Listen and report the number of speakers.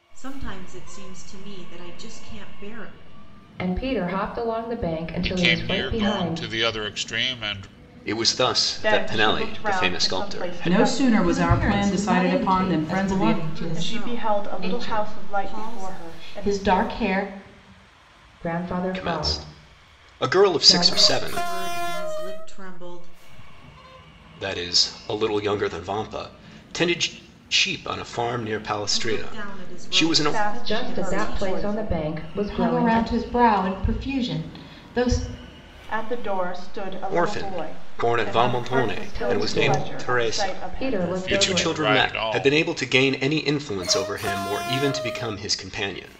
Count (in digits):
7